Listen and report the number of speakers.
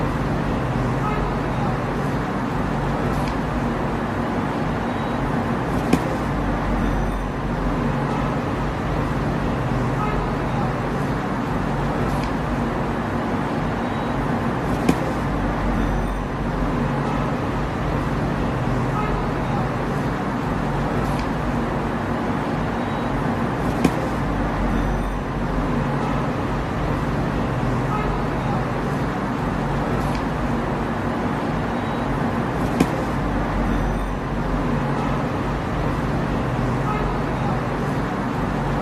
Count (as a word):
zero